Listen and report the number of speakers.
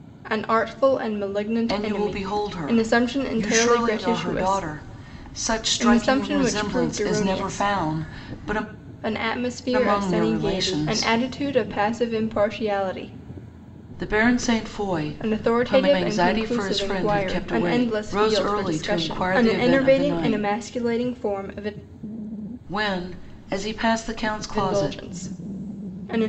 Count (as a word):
two